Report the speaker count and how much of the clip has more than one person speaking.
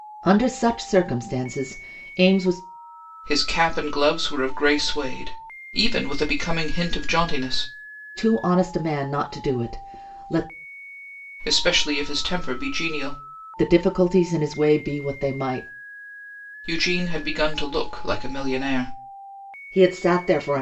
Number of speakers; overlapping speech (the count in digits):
2, no overlap